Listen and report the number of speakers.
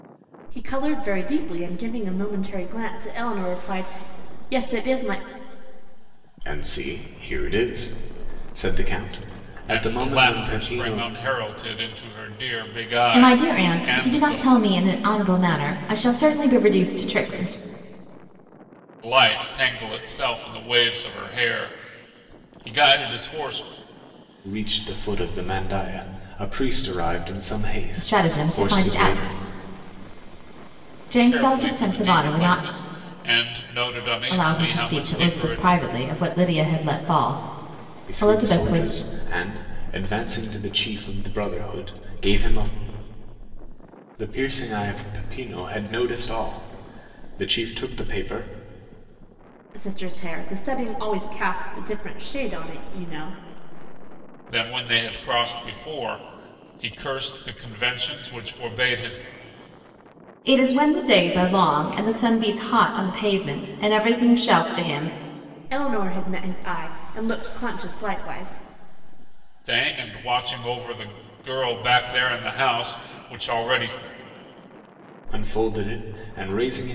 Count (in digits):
4